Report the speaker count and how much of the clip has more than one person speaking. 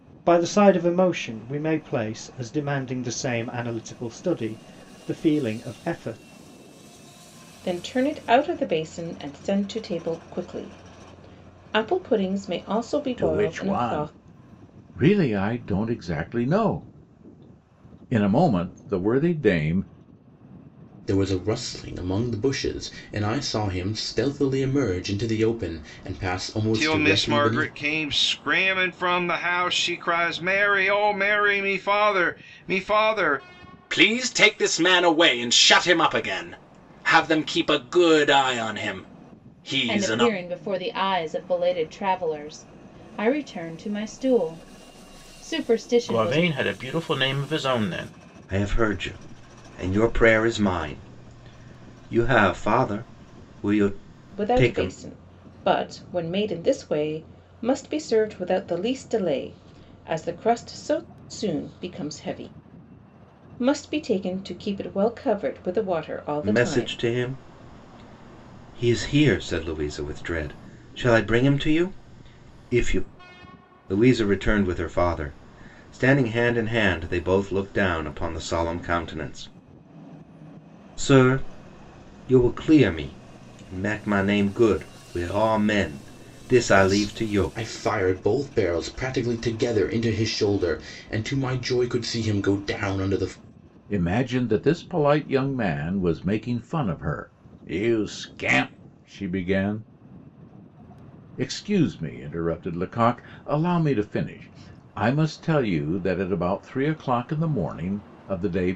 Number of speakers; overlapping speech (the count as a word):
nine, about 5%